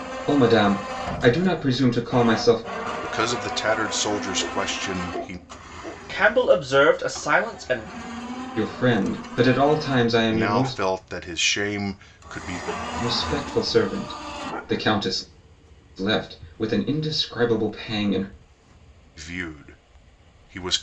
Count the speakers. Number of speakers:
three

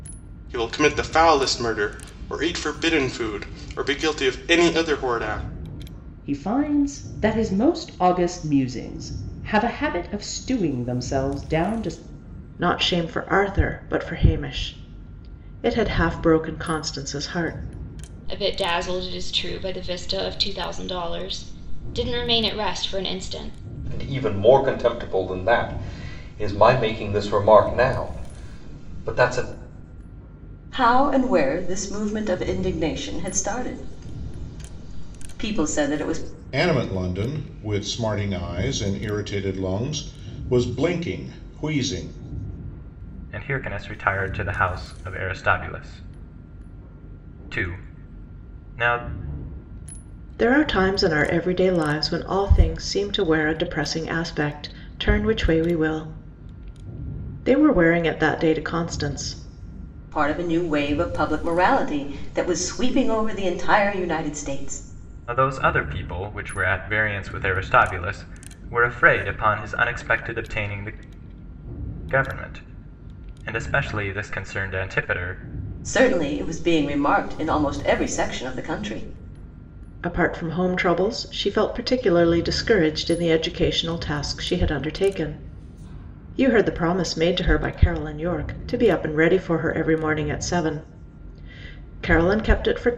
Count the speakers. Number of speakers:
eight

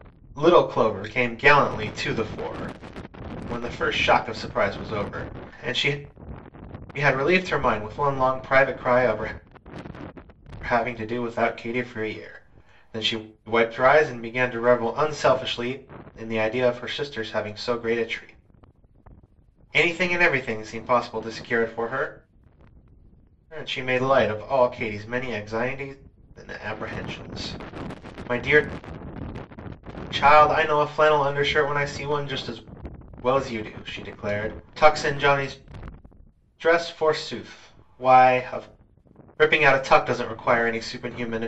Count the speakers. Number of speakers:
one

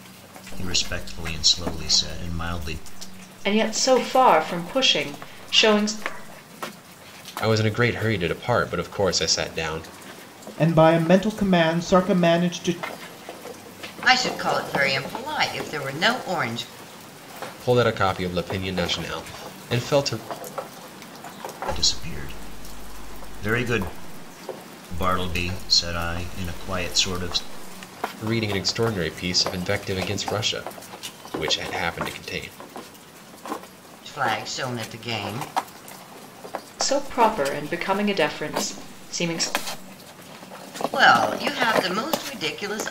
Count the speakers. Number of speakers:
five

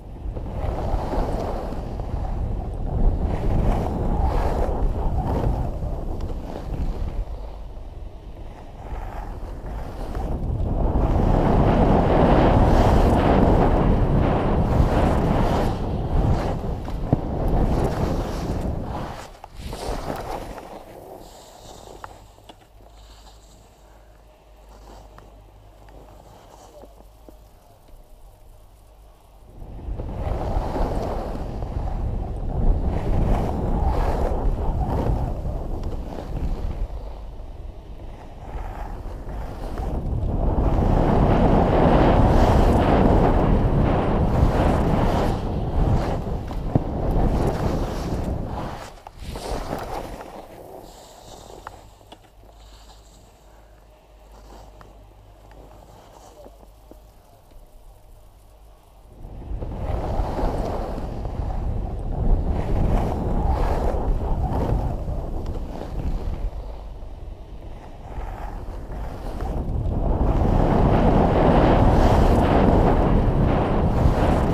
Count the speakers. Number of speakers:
zero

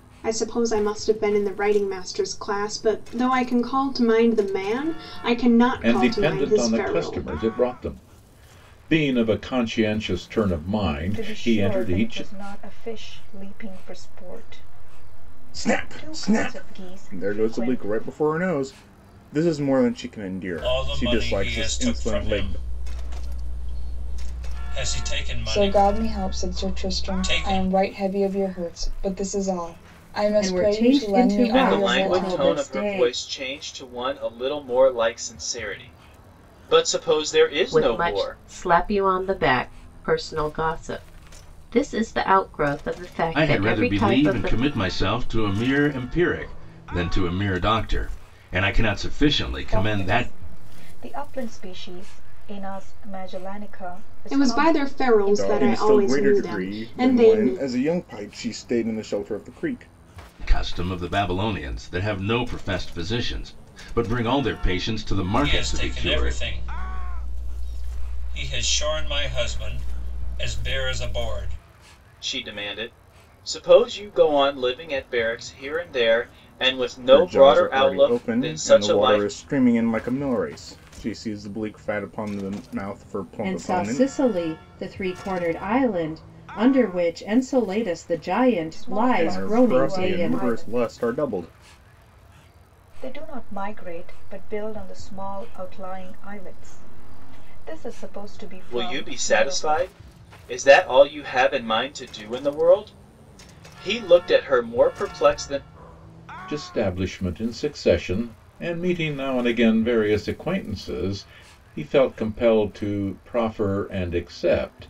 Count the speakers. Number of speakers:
ten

